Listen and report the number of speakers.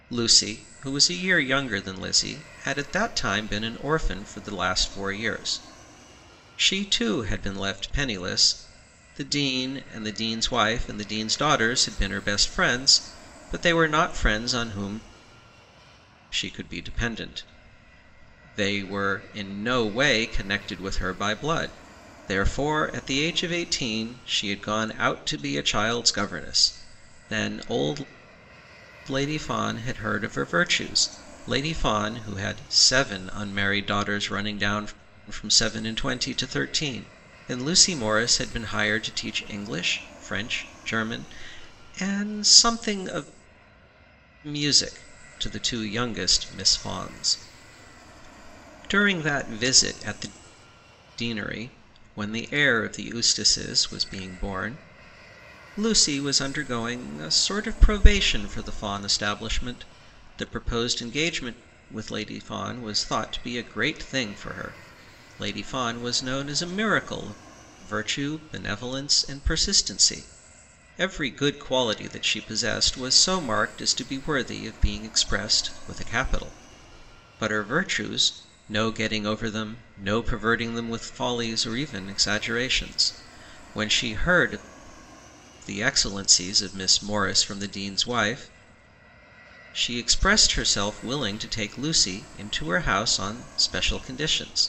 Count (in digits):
1